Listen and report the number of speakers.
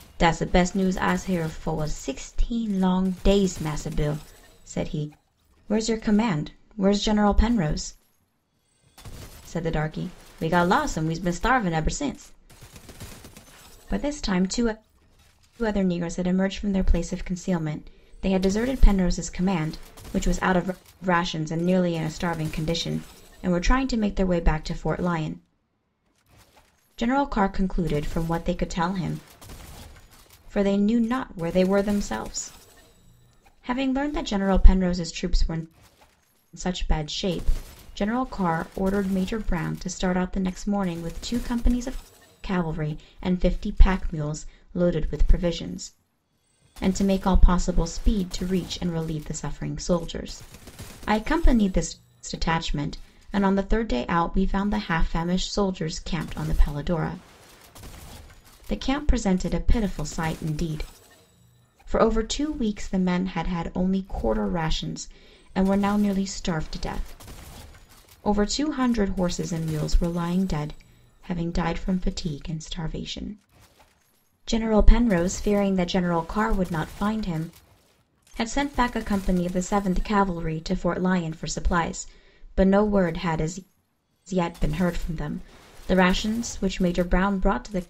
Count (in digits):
1